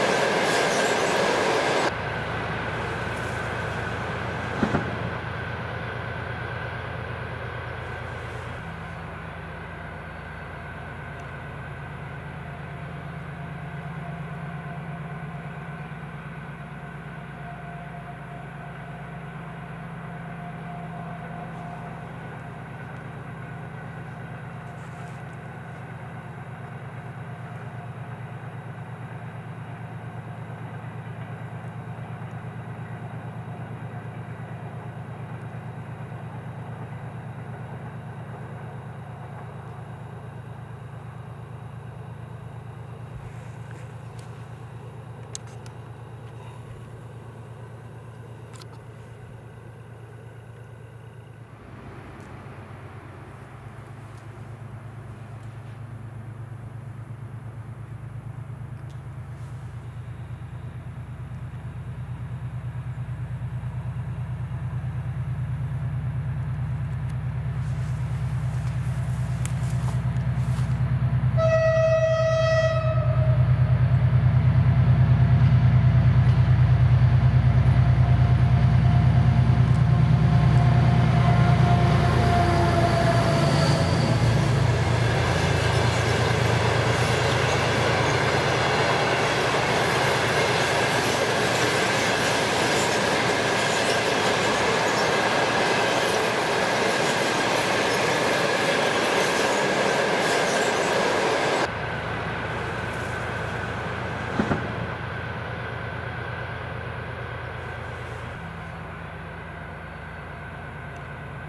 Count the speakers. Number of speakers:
0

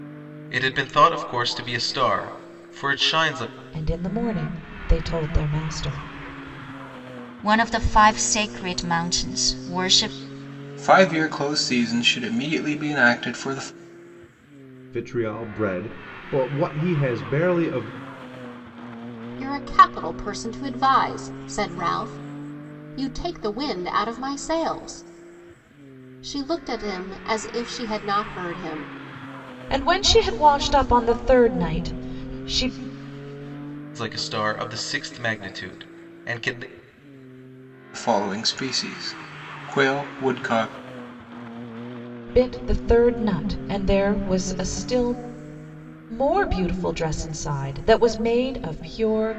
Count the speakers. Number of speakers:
6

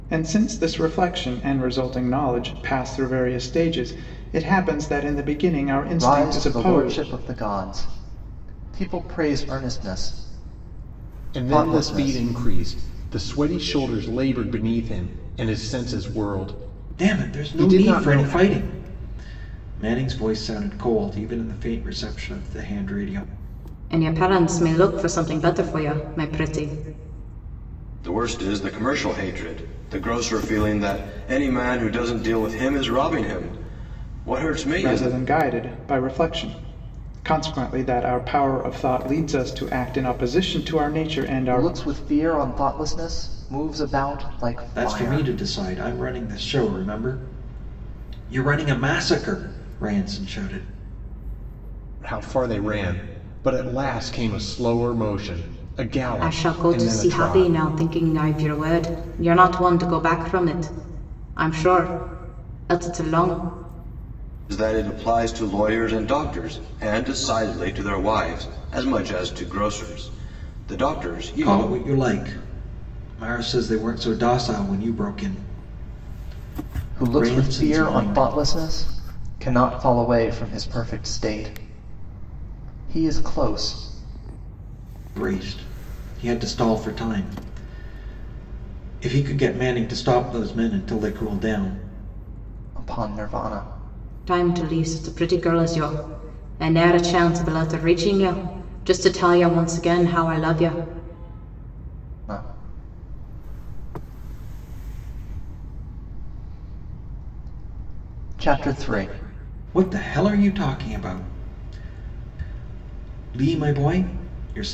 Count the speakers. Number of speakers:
6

